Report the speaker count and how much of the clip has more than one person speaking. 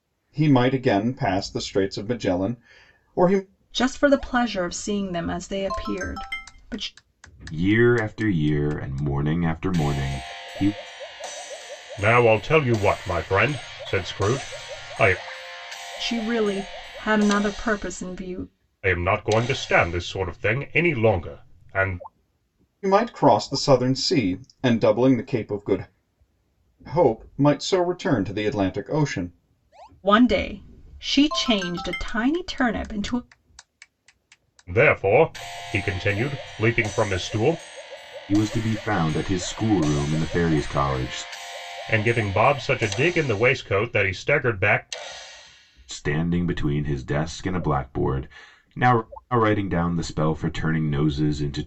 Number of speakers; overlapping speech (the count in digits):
4, no overlap